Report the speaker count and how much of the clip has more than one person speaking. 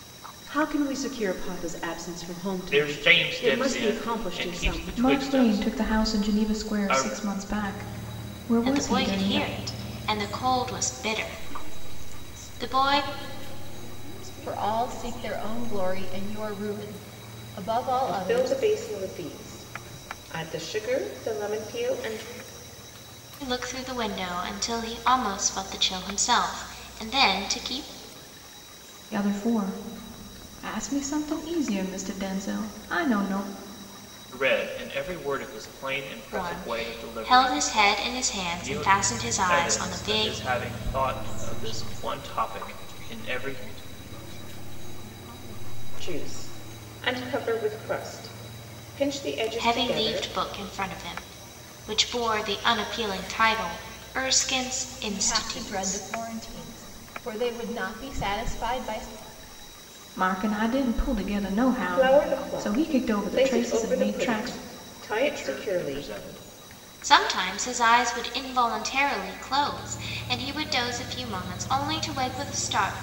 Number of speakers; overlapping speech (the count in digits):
7, about 28%